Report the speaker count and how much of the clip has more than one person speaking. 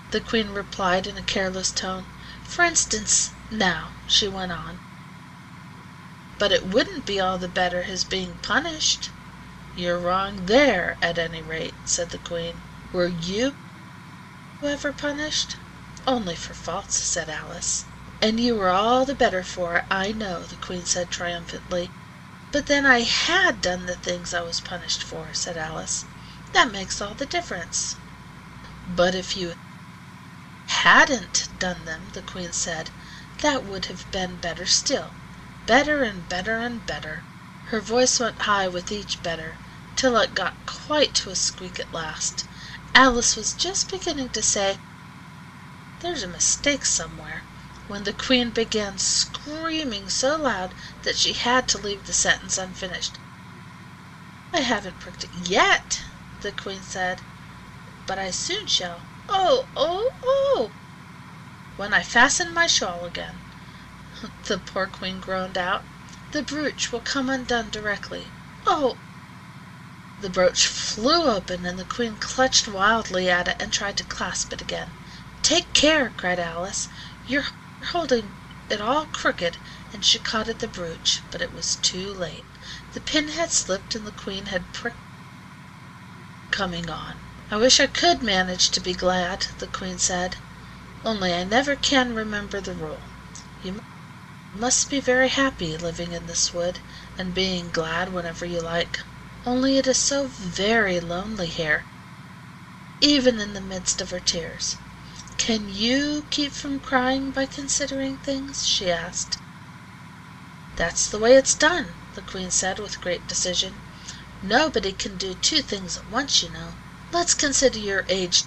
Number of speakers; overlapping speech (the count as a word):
one, no overlap